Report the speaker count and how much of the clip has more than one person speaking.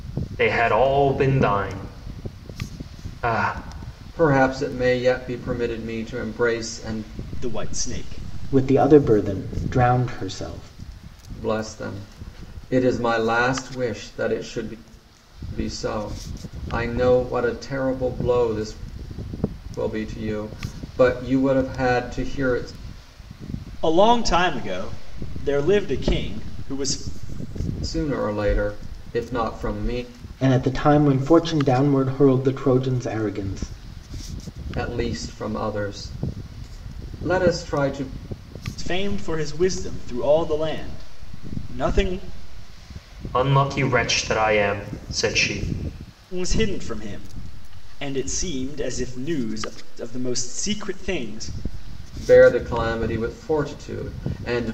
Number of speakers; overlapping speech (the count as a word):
four, no overlap